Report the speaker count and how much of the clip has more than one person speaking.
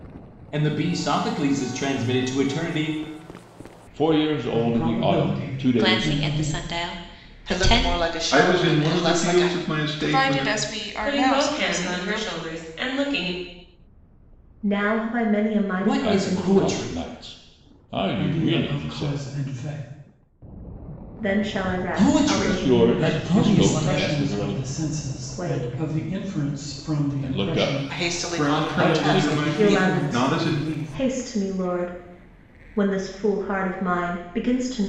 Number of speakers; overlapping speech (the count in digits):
9, about 44%